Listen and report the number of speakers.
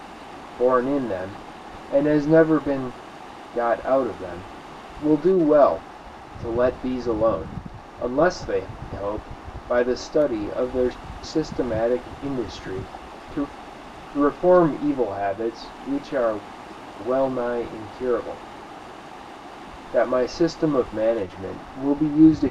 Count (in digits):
1